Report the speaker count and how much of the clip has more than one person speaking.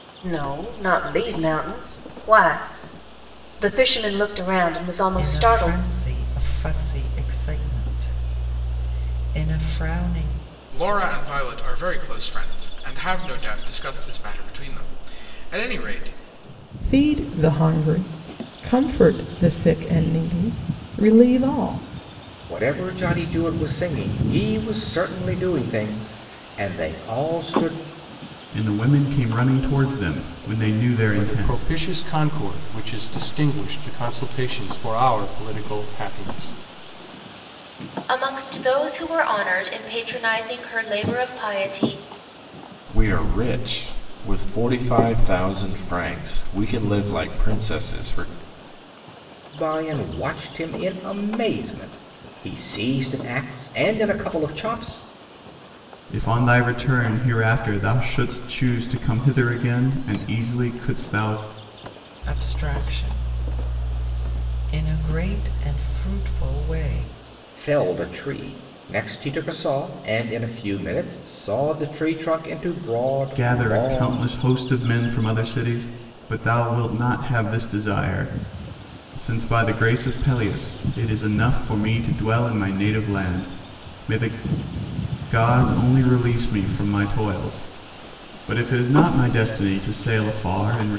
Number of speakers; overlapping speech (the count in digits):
9, about 3%